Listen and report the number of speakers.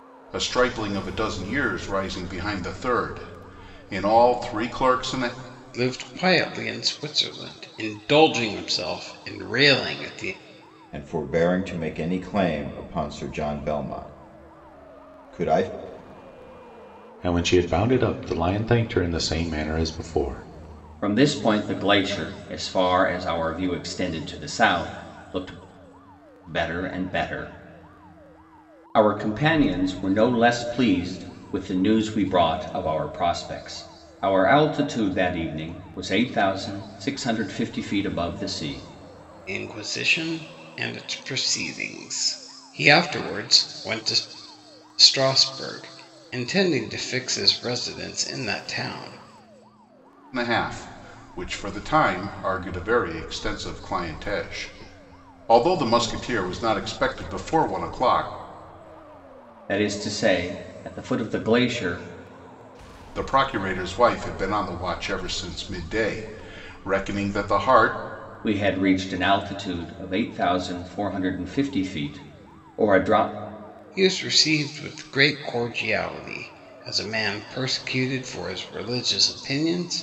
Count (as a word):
five